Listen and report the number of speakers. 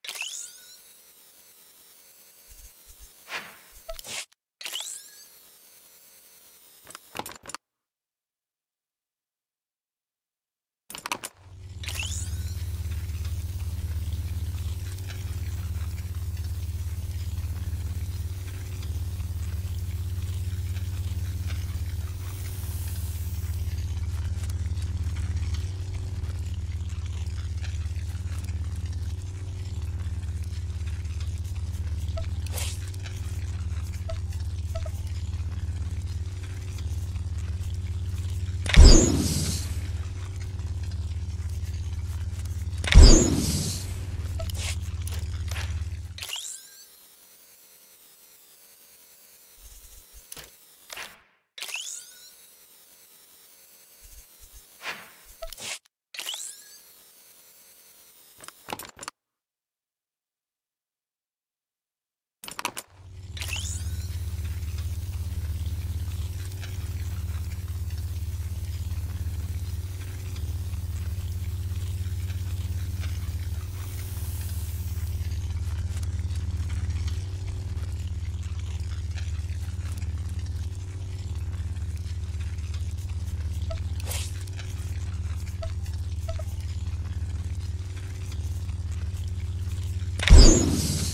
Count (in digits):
0